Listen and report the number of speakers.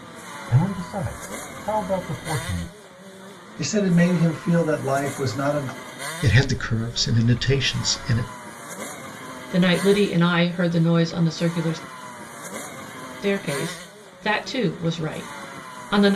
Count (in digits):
4